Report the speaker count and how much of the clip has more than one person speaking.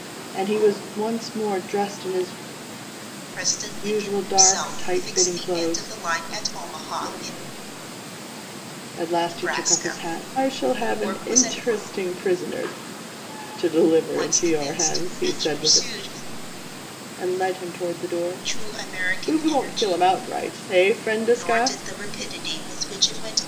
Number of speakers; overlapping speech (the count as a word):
two, about 36%